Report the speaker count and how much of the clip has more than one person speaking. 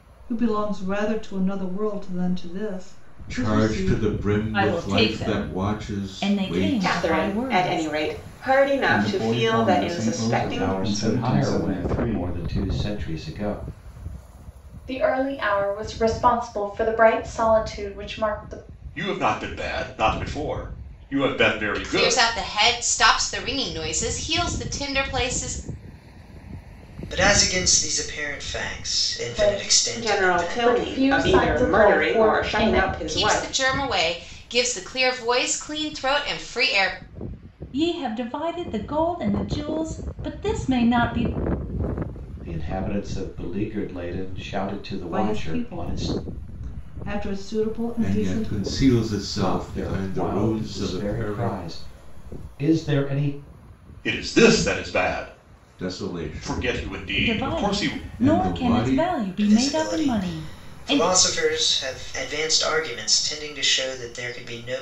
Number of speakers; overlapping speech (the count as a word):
ten, about 33%